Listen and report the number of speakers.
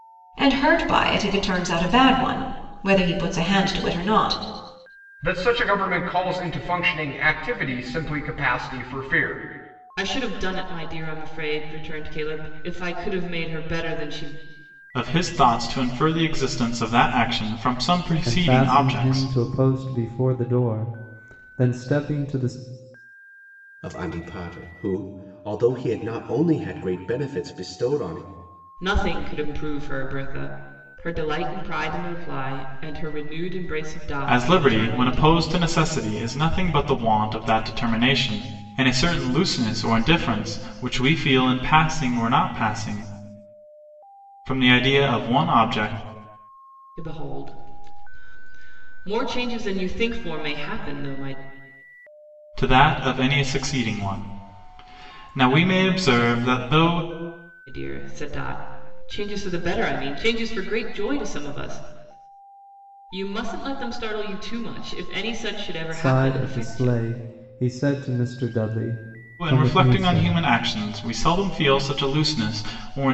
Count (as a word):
six